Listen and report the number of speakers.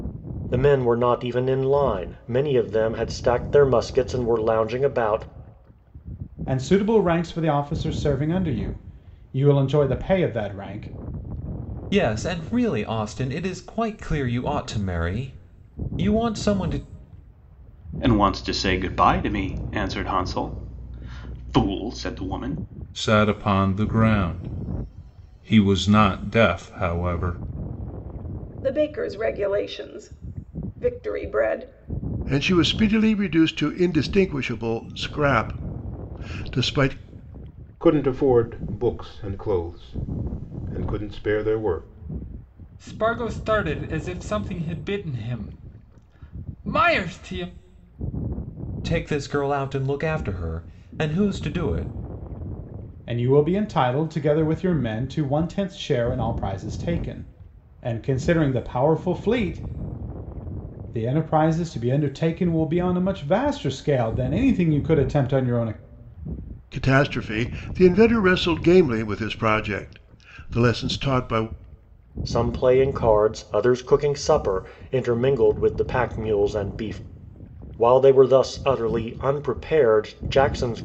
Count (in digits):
9